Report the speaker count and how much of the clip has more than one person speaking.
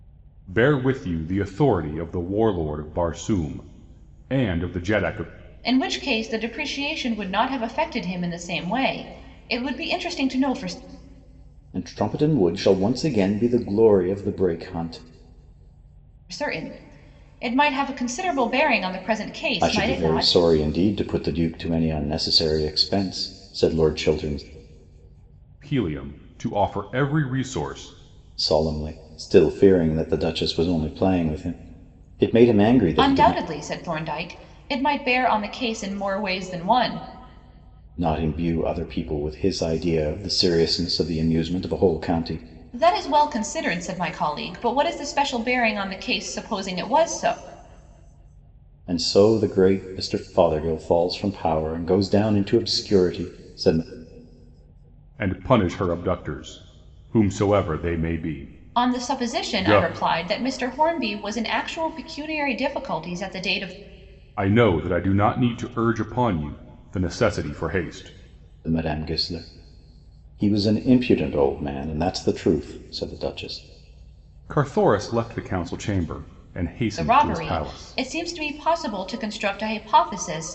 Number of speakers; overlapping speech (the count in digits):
3, about 4%